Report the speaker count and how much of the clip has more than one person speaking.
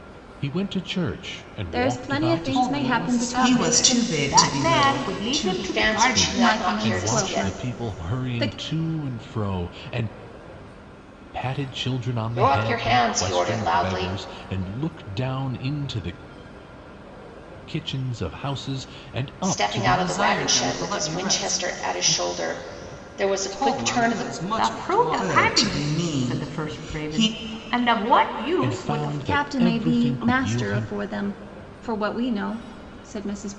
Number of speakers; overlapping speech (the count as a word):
six, about 52%